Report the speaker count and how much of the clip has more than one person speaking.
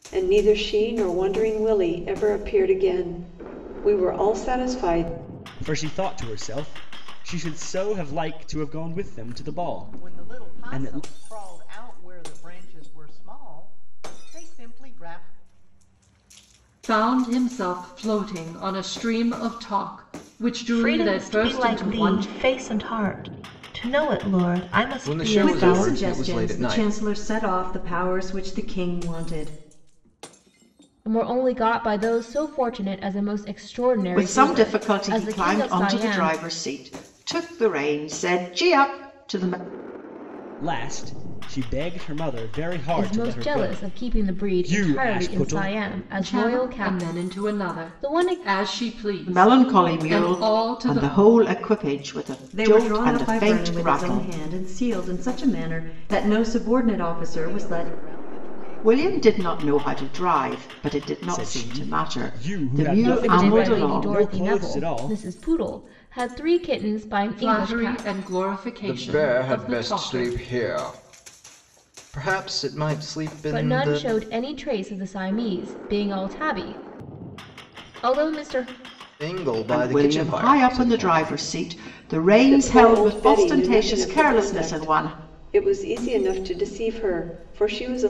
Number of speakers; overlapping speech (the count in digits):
9, about 33%